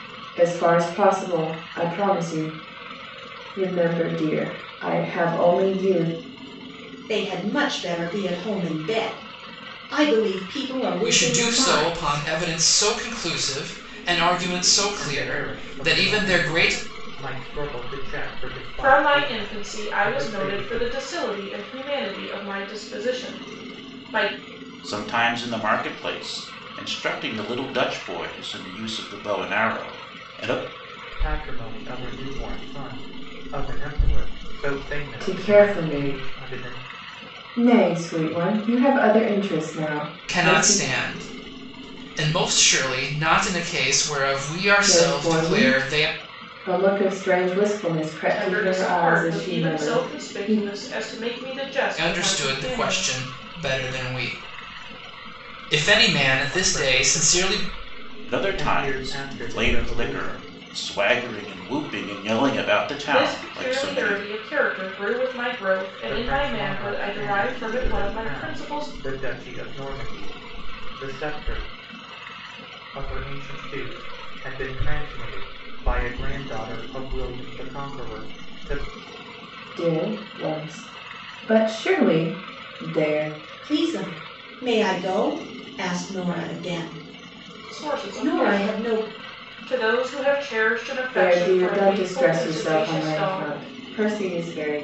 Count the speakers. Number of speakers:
6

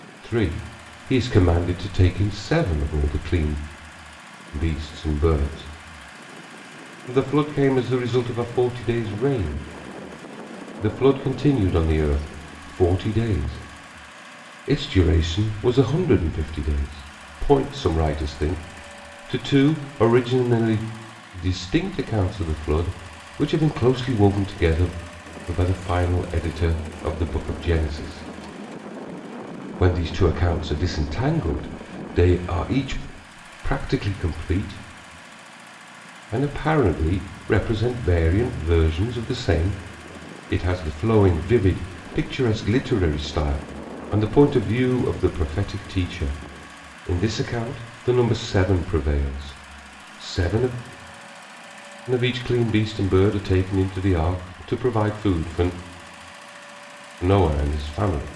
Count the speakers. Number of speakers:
1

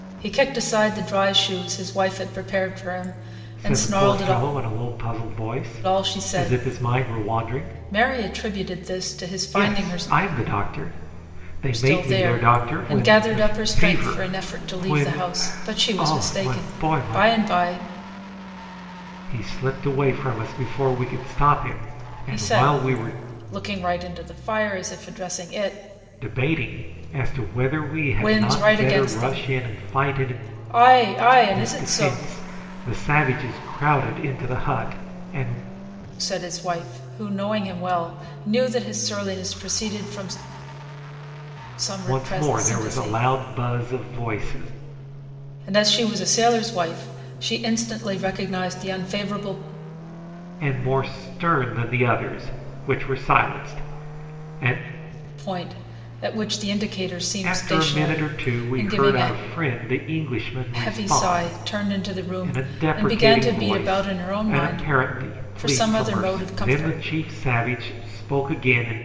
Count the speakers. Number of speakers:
2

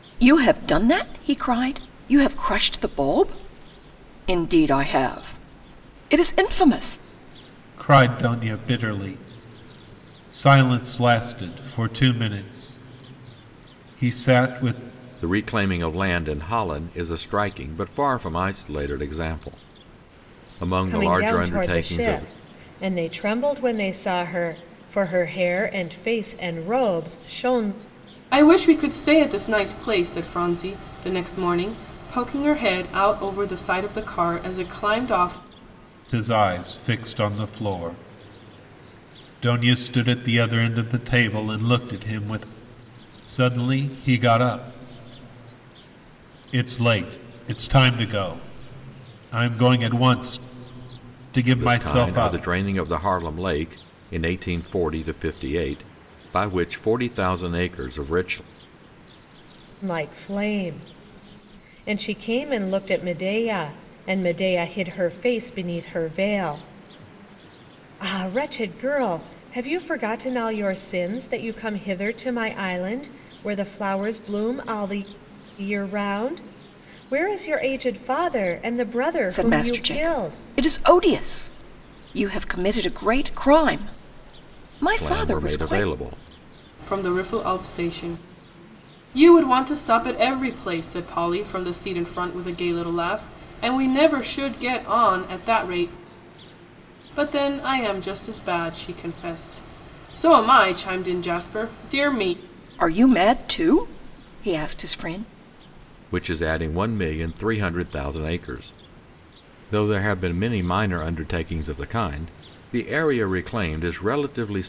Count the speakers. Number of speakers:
5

